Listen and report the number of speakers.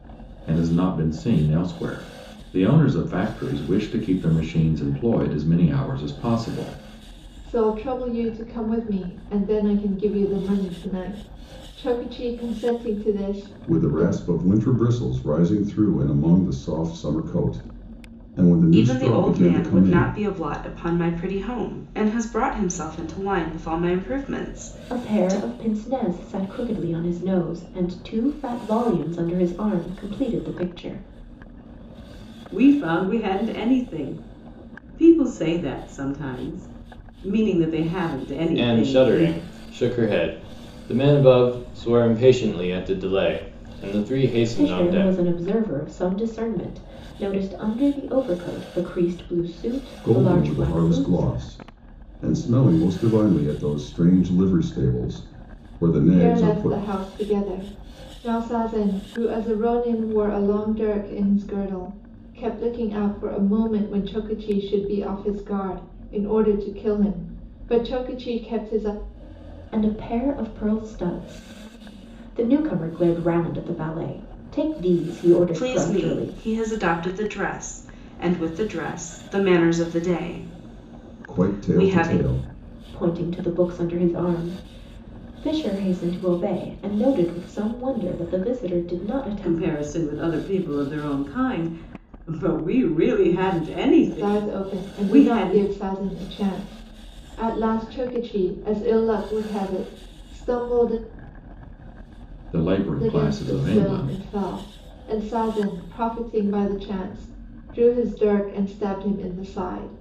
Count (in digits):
7